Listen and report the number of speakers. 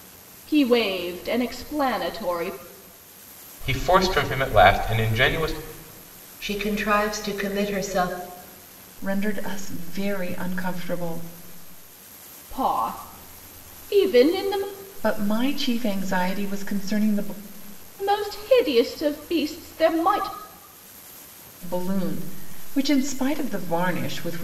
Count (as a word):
four